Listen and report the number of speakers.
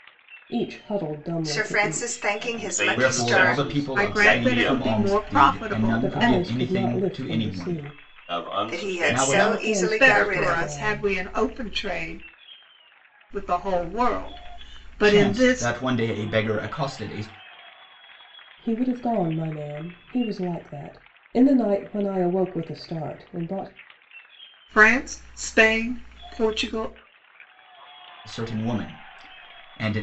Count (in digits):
5